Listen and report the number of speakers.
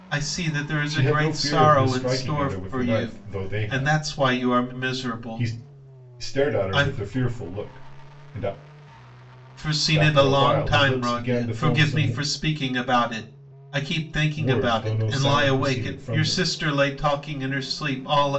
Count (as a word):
two